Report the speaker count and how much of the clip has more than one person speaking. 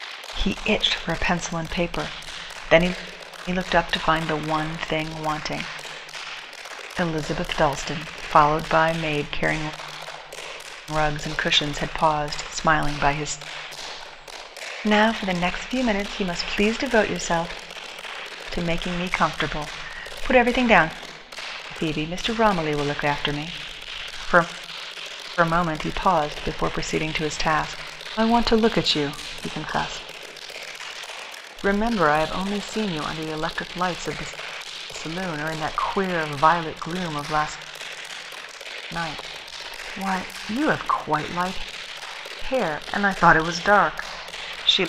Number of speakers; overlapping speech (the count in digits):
1, no overlap